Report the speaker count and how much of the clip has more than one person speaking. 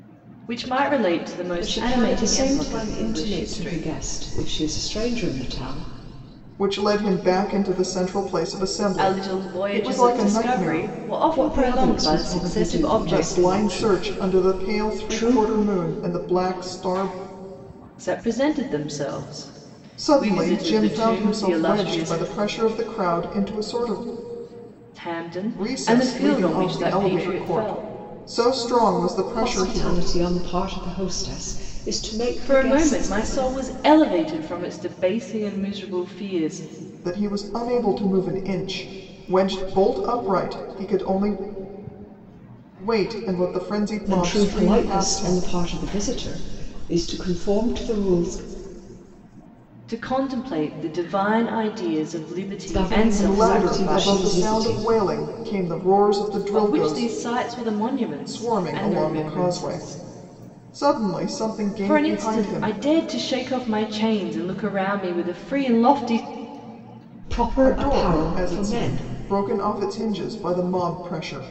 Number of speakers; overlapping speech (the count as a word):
three, about 32%